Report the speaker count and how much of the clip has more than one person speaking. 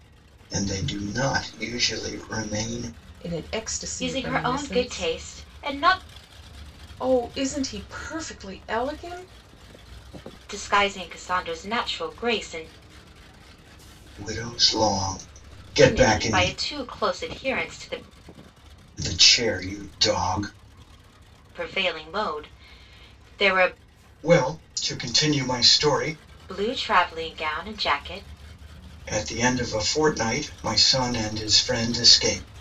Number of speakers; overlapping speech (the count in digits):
3, about 6%